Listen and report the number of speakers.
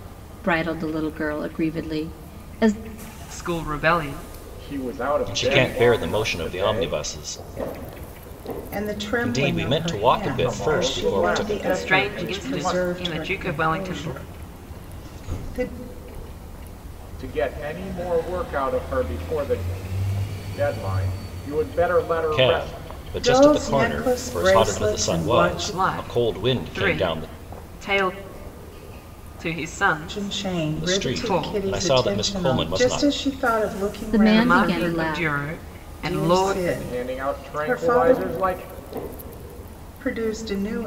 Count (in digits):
5